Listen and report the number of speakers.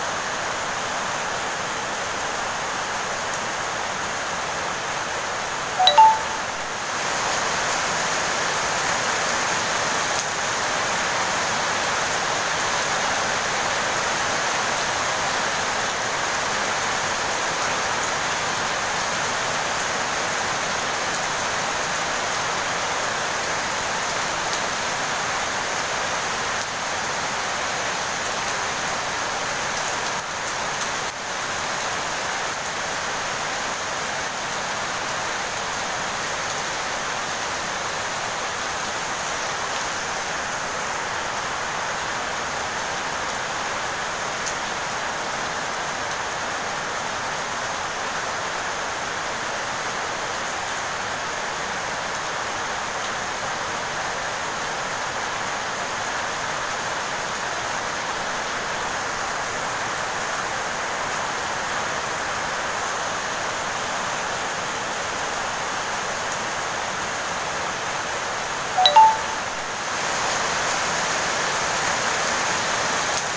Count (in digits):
0